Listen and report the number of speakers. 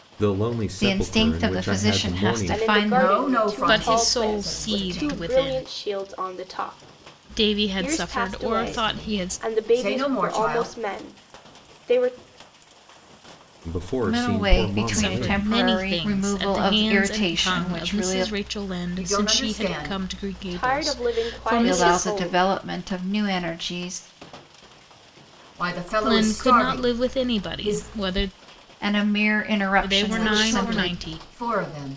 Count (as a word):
five